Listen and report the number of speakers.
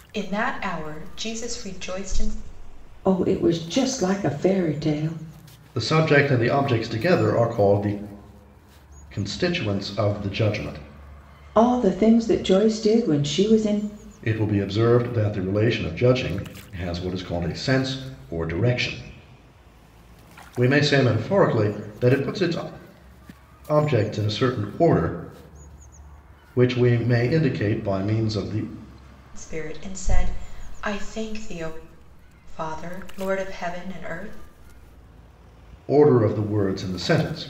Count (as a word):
three